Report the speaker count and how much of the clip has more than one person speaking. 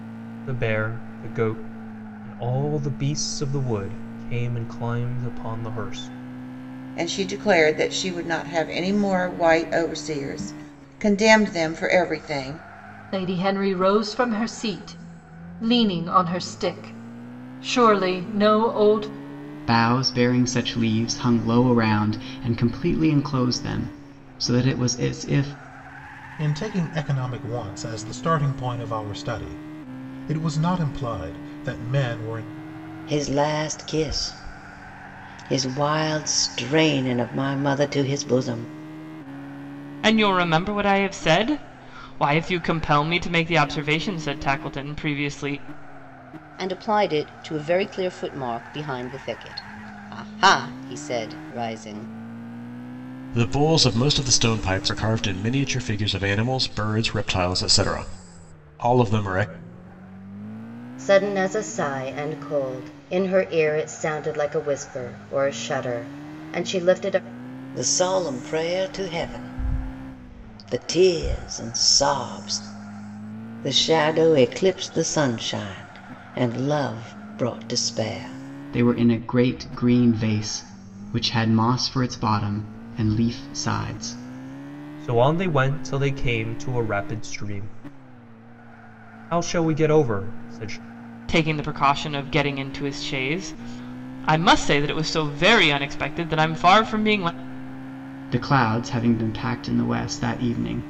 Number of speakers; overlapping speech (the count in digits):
10, no overlap